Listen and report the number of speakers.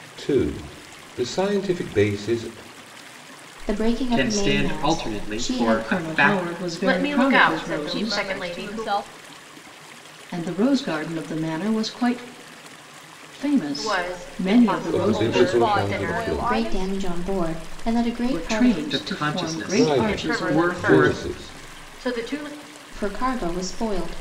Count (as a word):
six